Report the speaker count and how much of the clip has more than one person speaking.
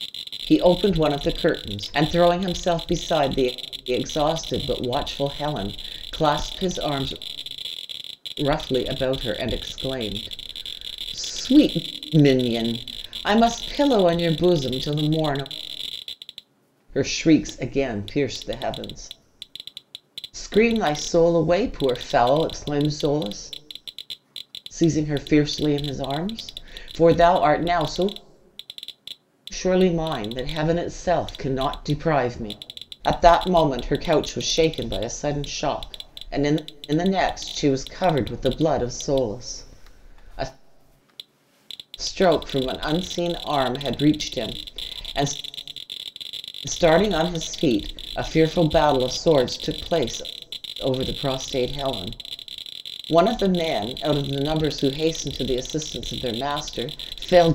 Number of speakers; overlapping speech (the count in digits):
1, no overlap